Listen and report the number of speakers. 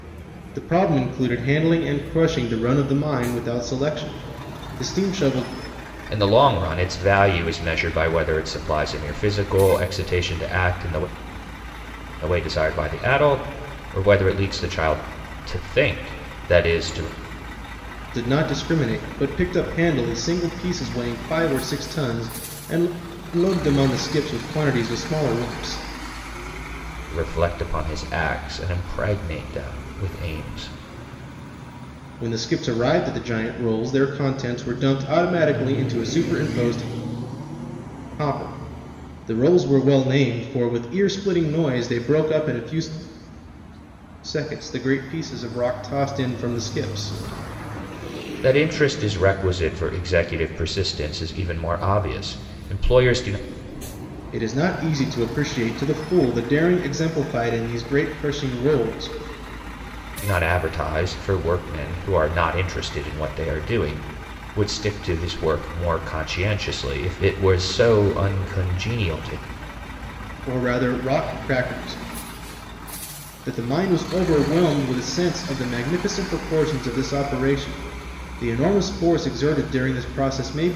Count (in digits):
2